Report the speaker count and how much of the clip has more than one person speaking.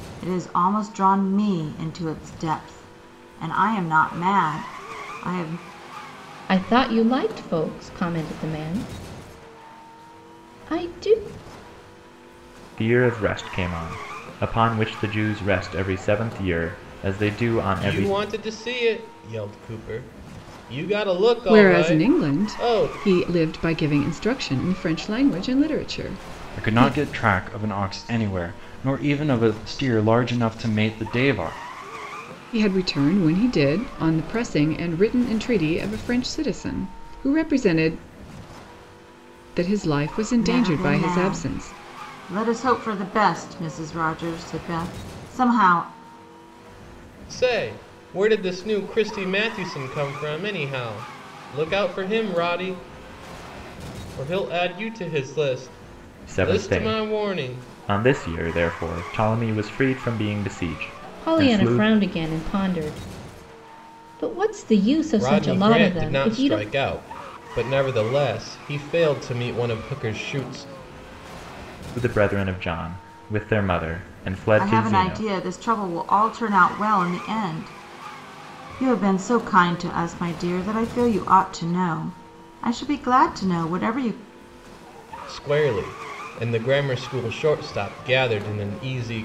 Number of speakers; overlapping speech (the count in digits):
6, about 9%